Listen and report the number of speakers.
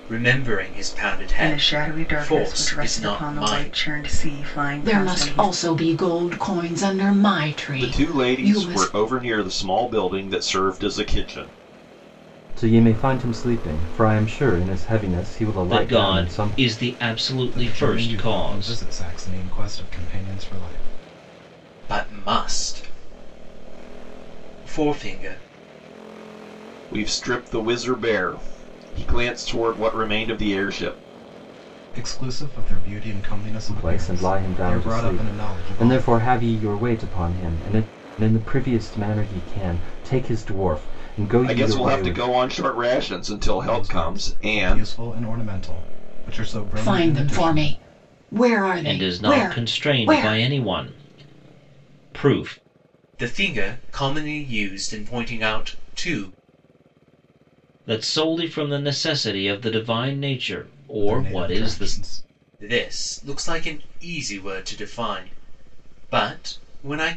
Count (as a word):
seven